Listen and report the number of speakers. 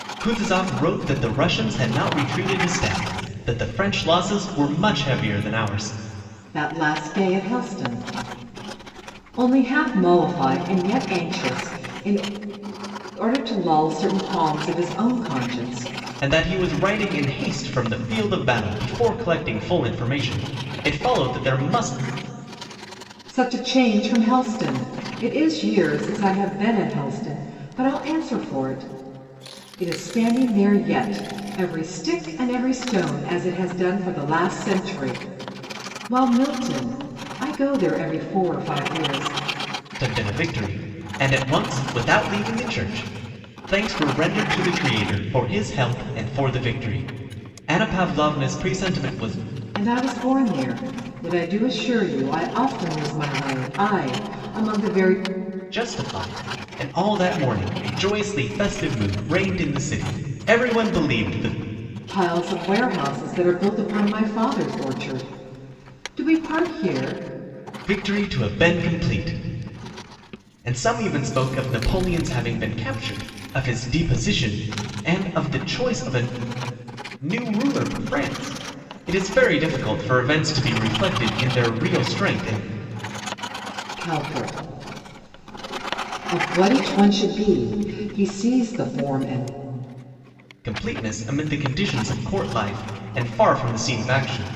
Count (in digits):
2